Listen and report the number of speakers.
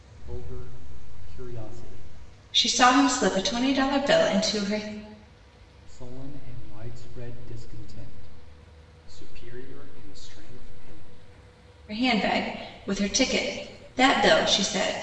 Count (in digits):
2